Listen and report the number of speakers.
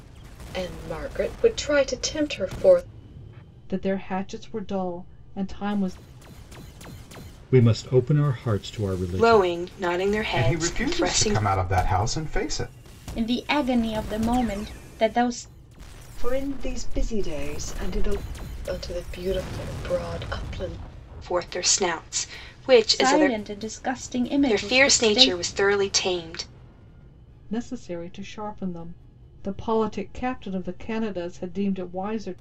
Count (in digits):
7